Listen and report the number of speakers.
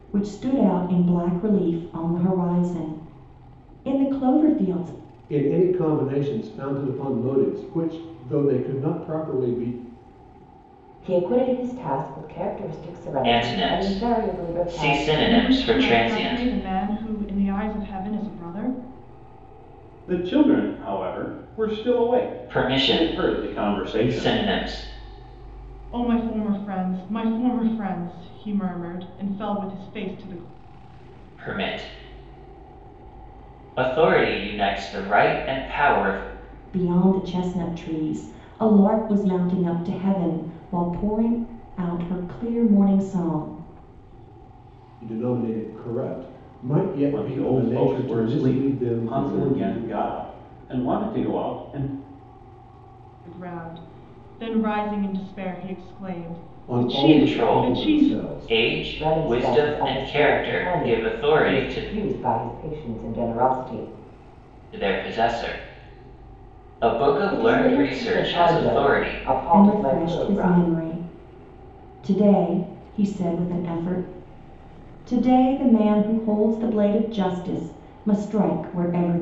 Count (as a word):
six